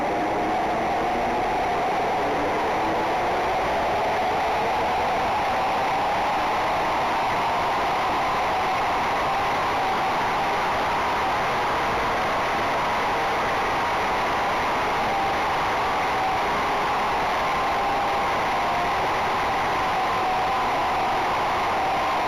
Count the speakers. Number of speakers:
0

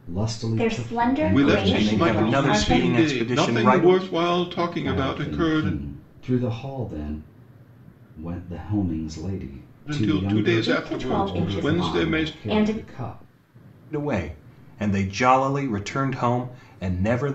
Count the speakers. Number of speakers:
4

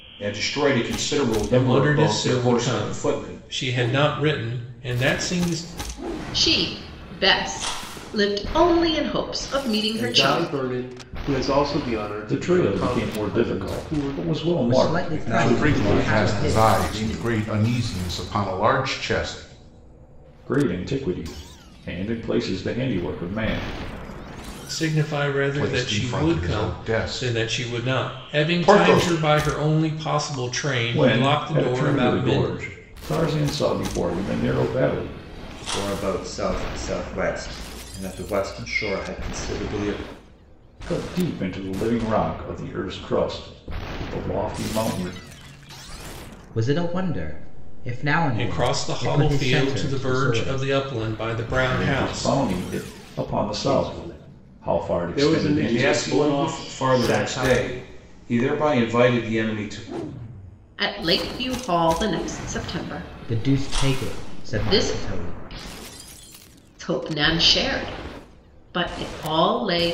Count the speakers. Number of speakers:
8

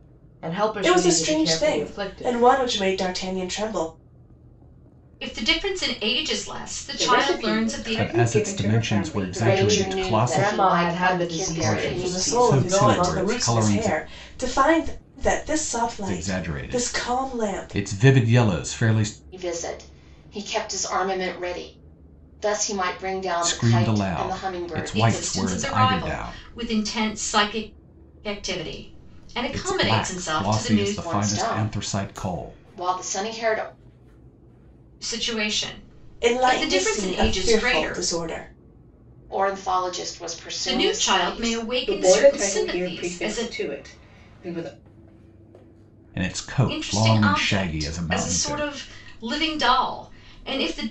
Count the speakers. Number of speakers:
6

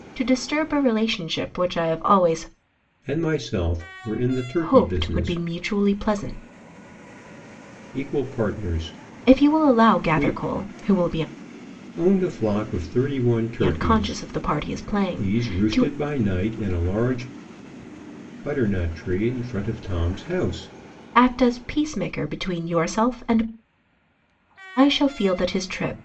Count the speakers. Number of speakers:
2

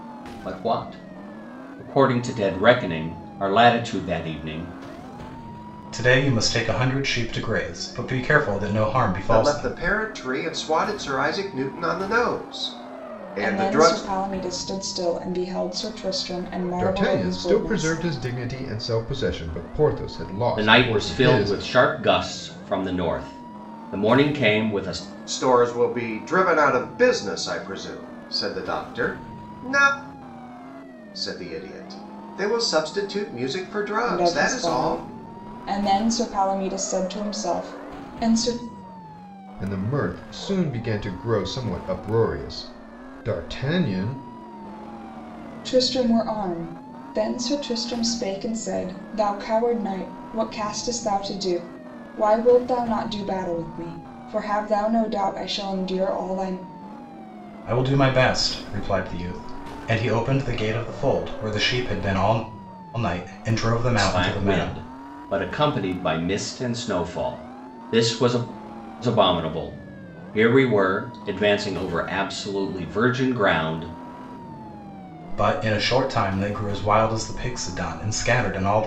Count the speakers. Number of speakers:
5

